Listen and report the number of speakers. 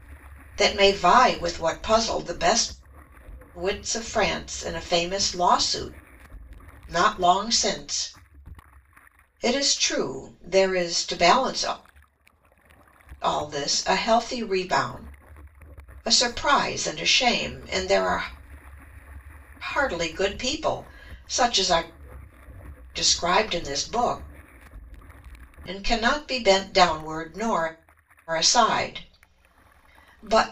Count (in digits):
1